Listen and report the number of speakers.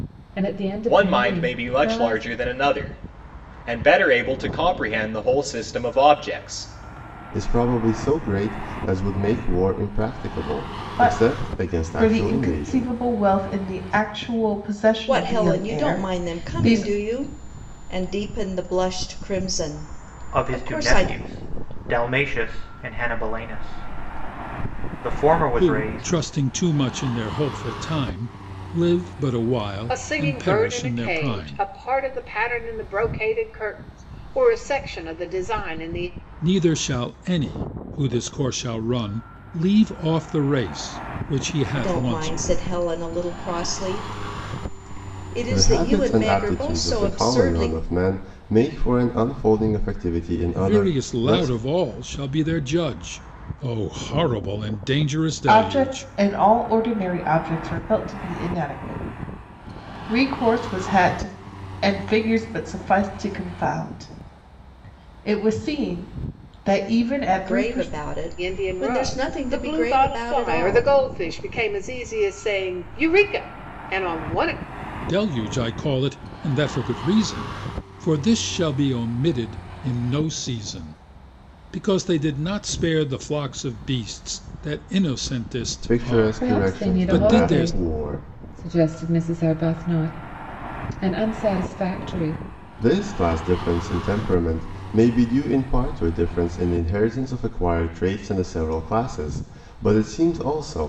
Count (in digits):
8